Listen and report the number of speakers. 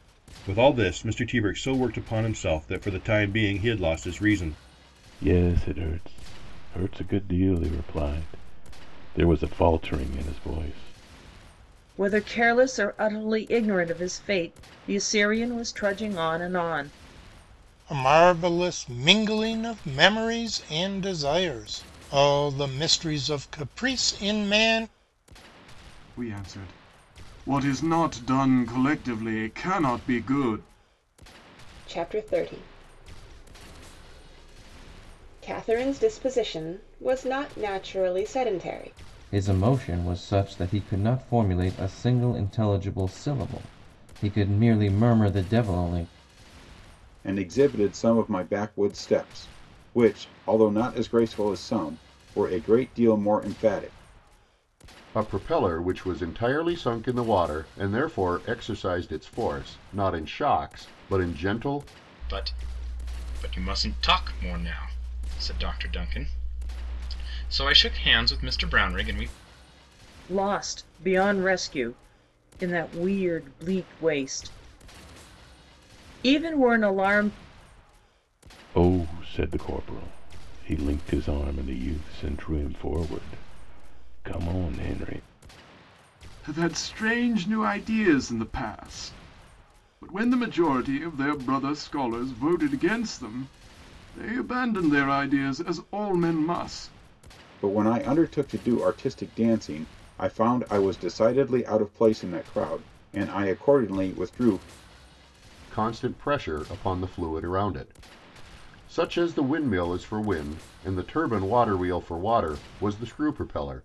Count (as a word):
ten